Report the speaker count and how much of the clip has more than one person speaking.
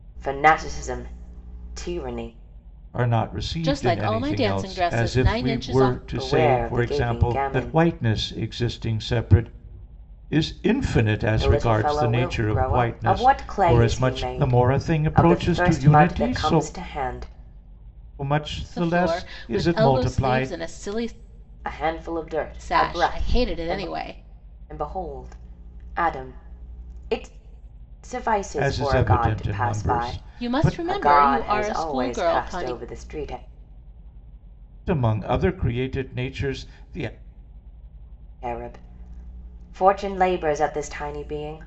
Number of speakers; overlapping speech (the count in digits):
3, about 40%